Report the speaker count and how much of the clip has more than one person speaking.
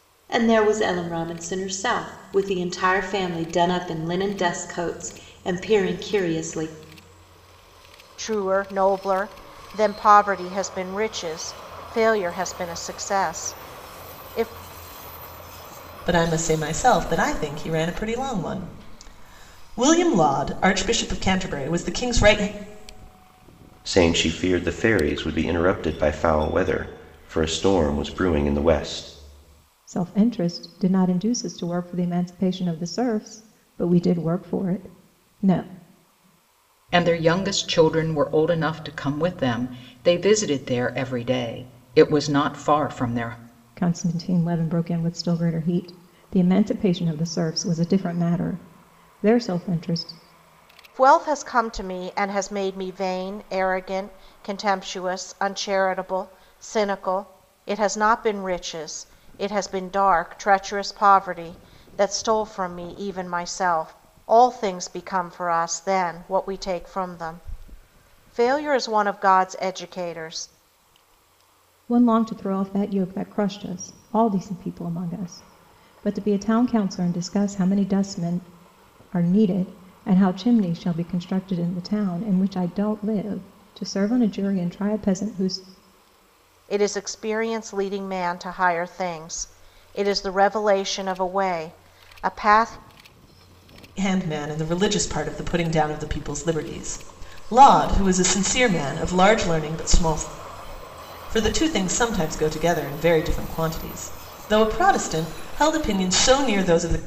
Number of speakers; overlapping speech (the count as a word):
six, no overlap